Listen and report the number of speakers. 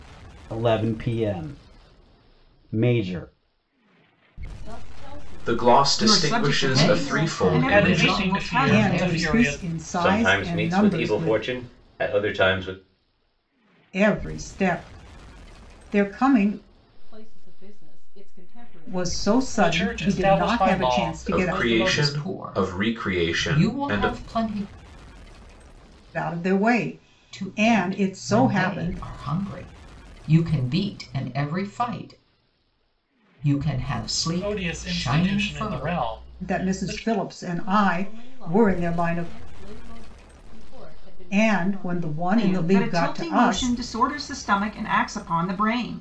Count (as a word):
eight